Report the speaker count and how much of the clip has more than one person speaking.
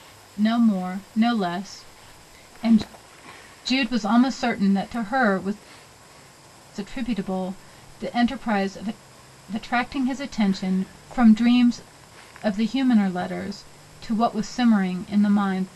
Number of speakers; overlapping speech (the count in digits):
1, no overlap